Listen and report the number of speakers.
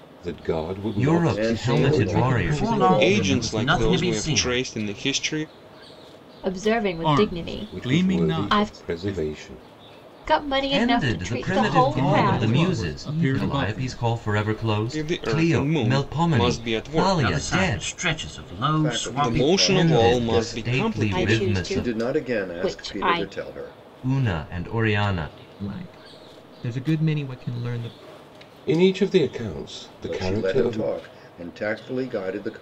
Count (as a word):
eight